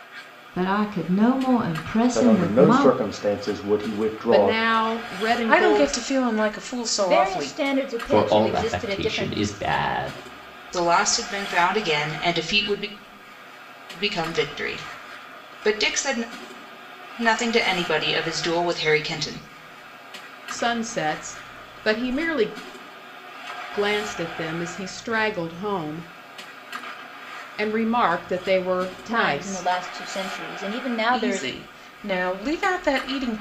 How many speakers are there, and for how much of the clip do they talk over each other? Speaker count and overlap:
7, about 14%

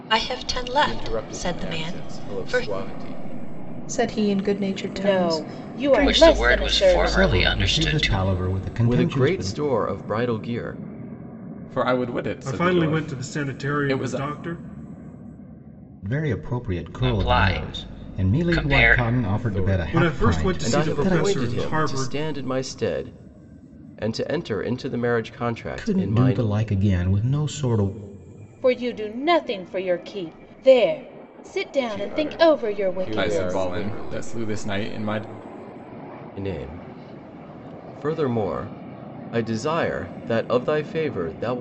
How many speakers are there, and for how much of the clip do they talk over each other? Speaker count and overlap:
9, about 38%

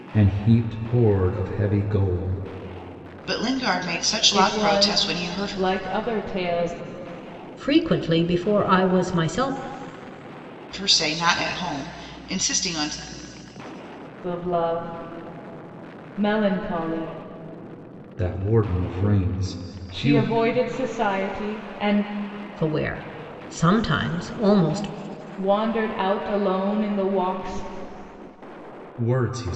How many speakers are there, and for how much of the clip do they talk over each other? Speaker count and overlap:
4, about 6%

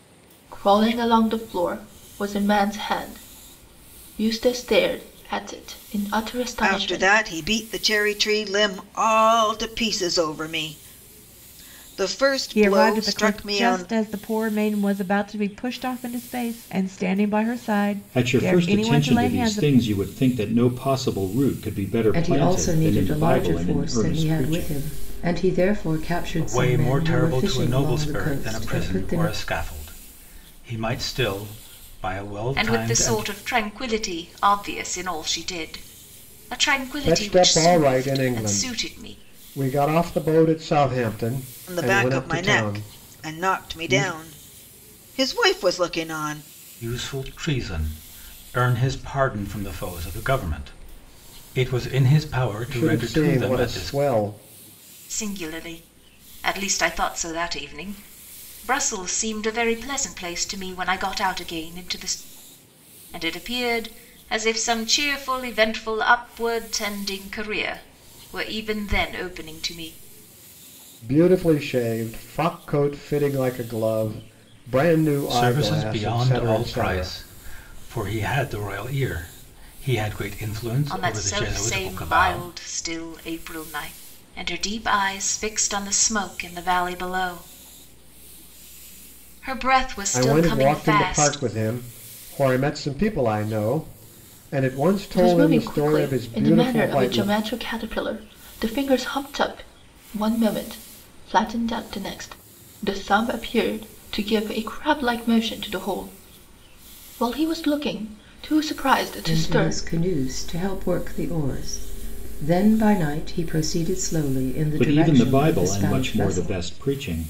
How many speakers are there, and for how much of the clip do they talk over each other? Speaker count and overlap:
8, about 22%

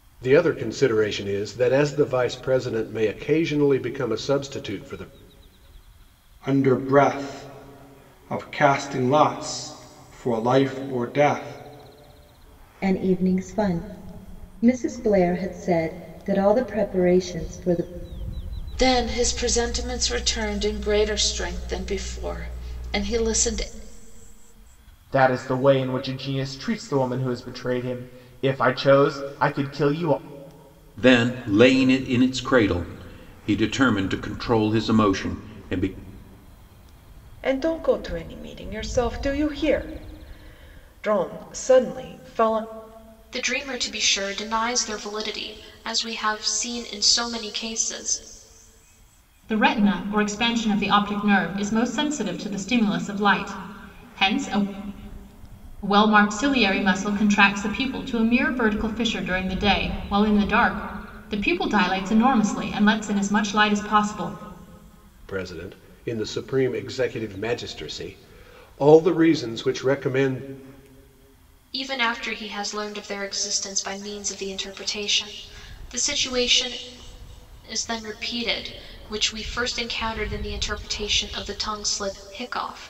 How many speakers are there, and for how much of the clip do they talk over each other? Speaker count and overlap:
9, no overlap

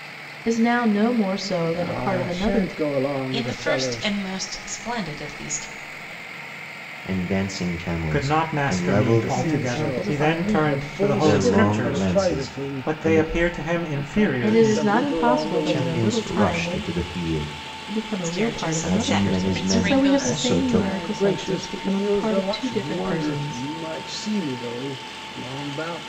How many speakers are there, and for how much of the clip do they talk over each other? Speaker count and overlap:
5, about 60%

